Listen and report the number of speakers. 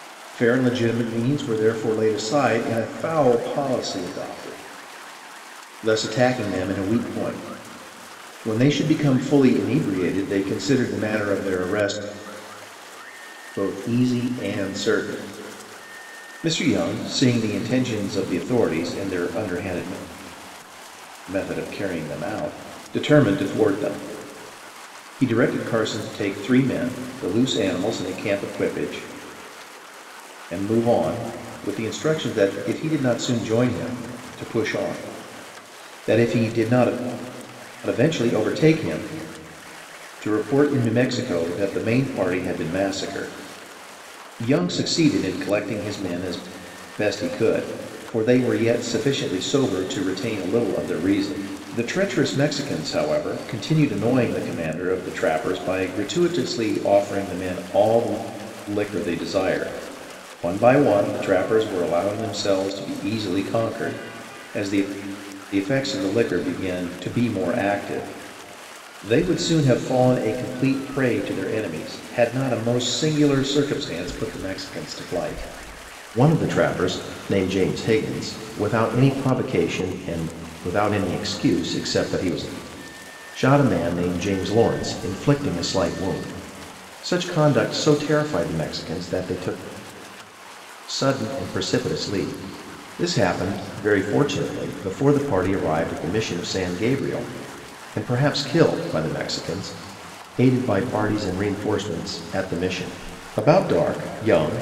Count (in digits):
1